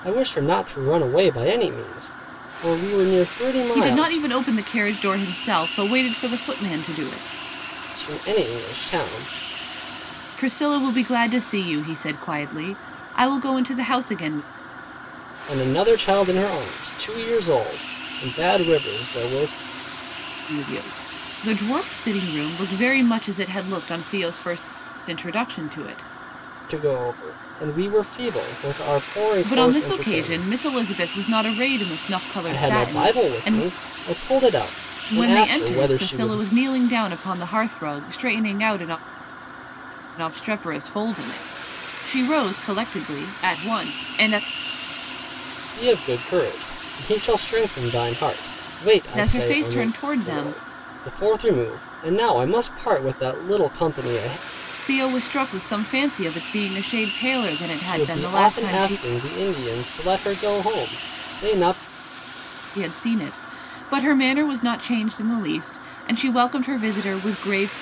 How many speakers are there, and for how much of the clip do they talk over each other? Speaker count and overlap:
two, about 10%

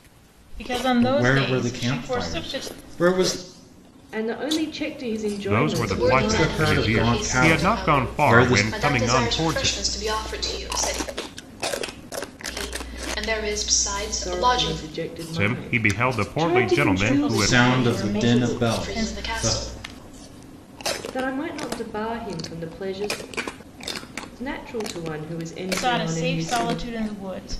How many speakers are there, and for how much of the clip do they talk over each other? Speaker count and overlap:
five, about 42%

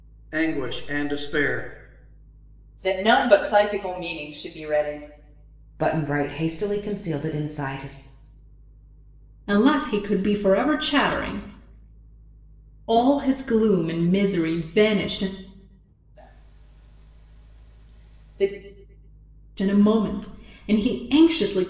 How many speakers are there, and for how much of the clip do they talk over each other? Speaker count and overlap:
four, no overlap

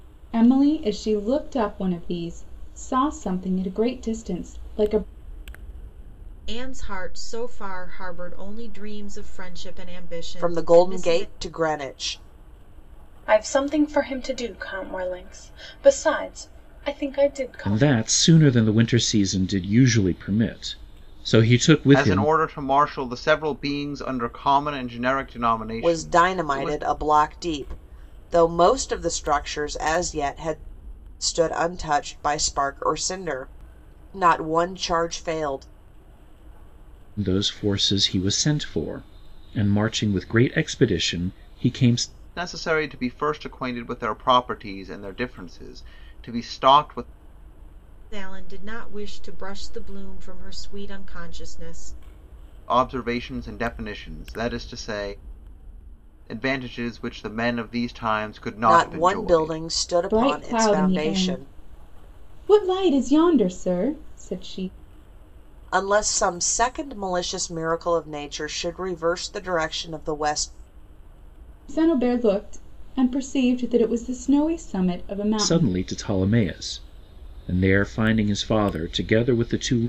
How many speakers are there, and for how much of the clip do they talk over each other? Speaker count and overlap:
six, about 7%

